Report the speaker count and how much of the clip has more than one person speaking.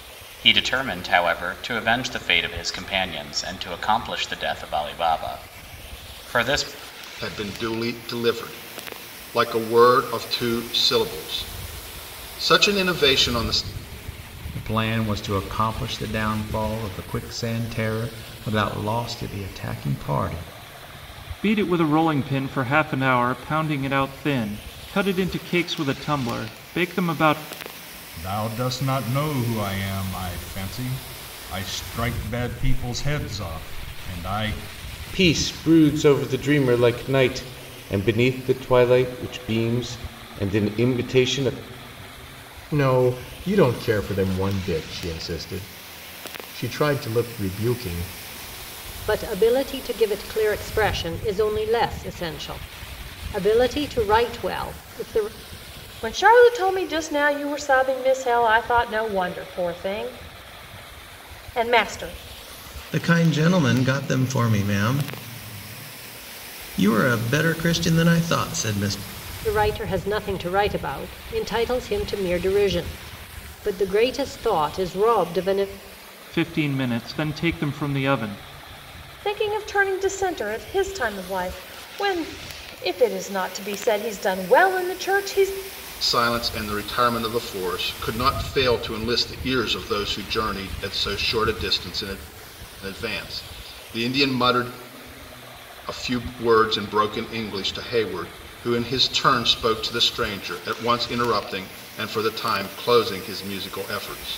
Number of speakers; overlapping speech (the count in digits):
10, no overlap